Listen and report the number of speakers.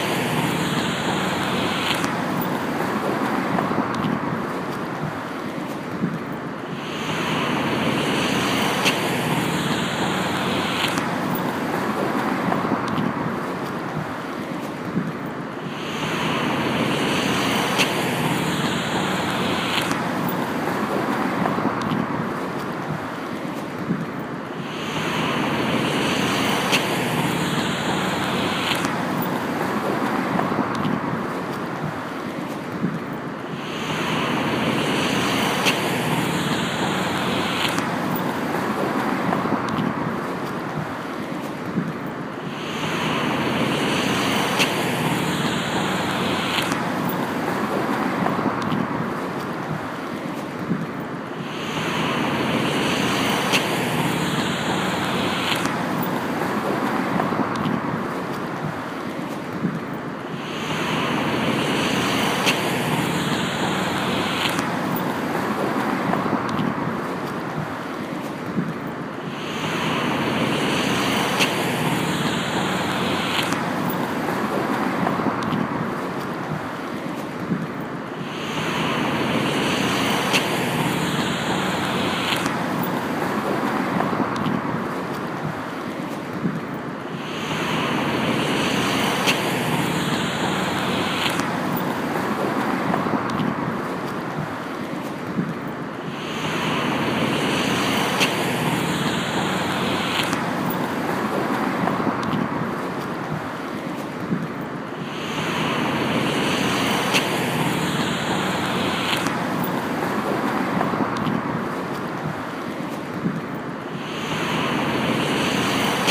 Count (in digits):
0